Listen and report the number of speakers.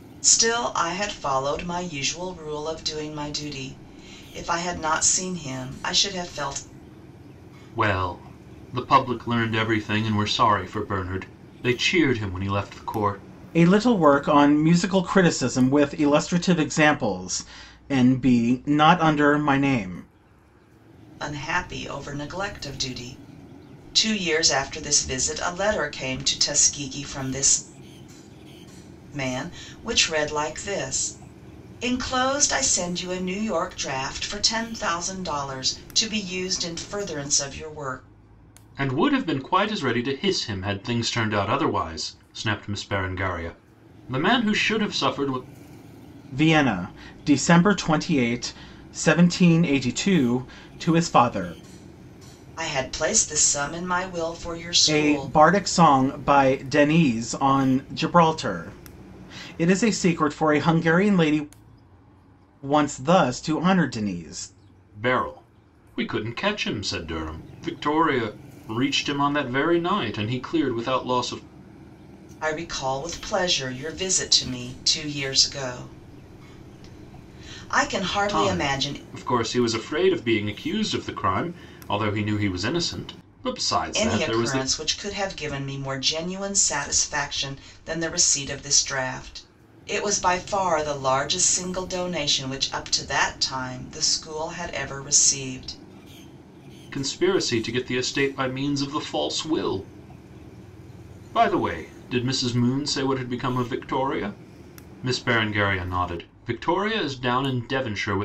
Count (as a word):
three